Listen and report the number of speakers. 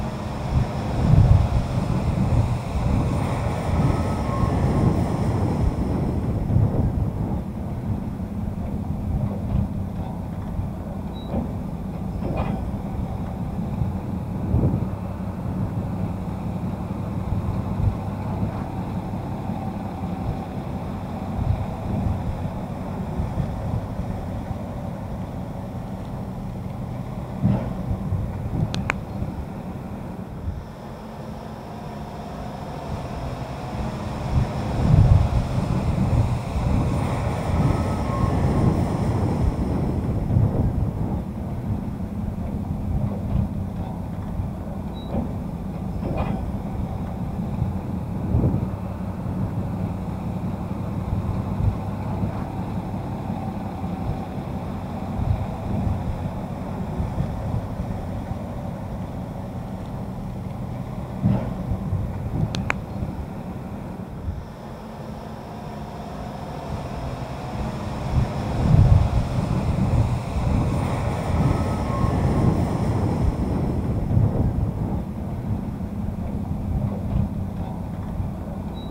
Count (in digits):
0